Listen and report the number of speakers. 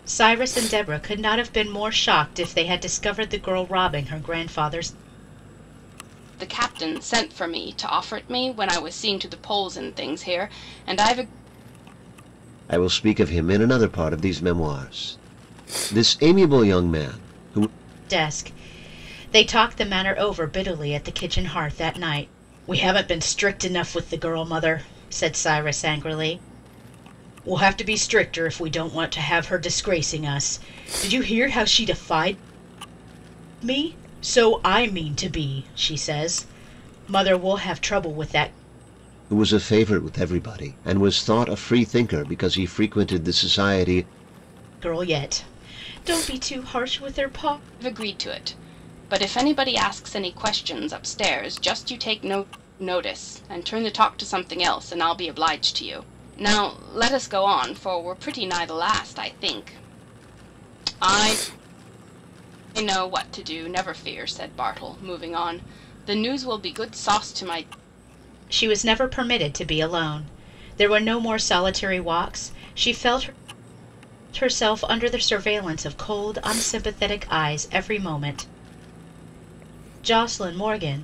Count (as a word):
three